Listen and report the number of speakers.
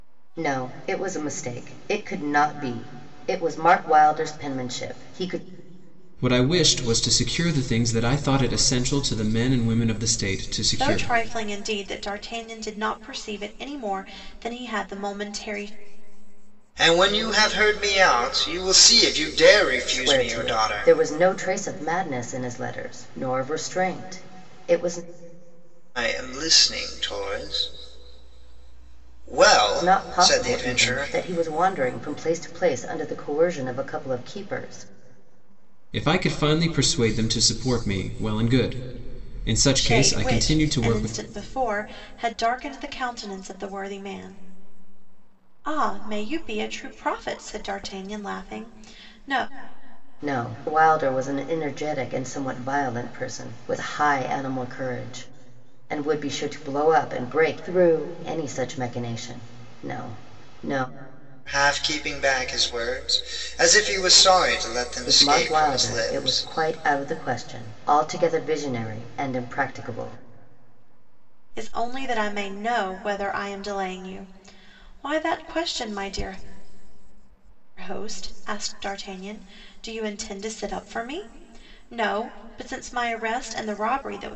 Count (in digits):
4